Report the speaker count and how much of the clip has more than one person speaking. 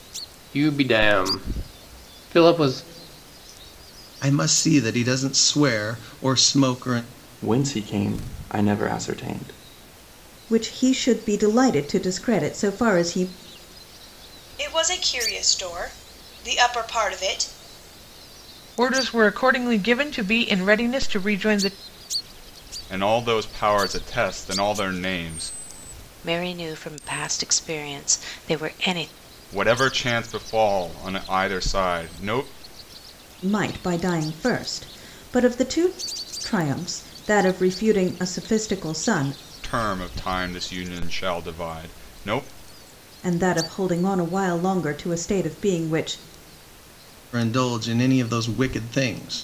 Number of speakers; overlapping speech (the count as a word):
eight, no overlap